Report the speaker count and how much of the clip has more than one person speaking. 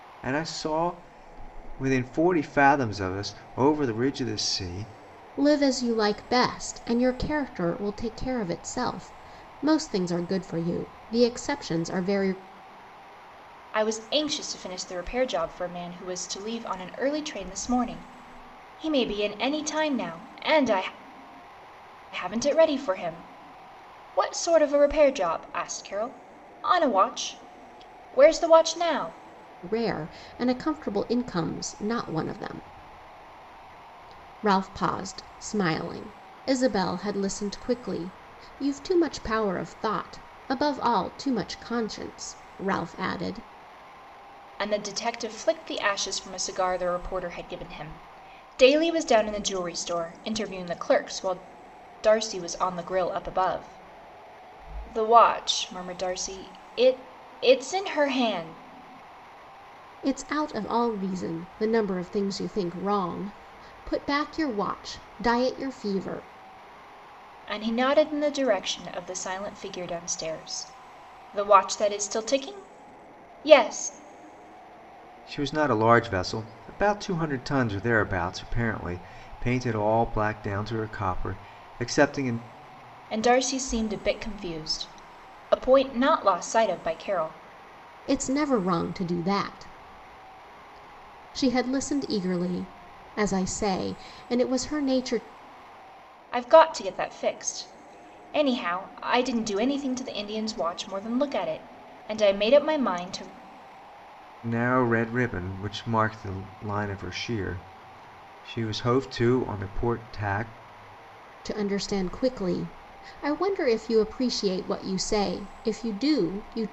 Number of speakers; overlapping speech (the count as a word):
three, no overlap